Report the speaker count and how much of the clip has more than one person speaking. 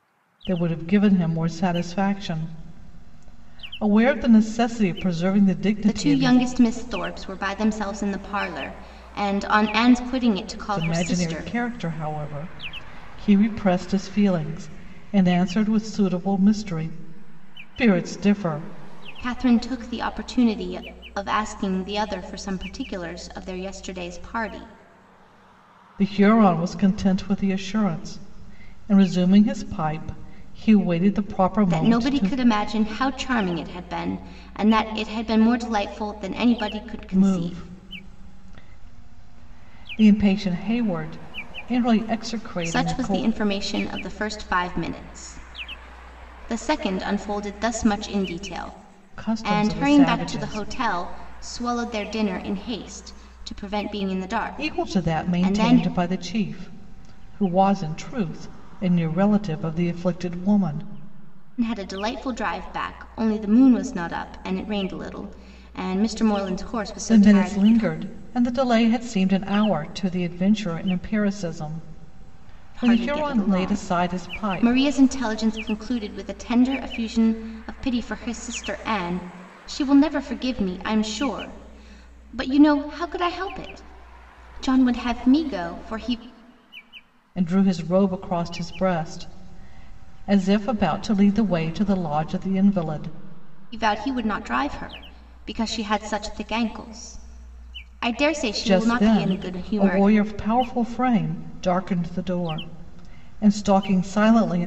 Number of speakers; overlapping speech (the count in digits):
2, about 9%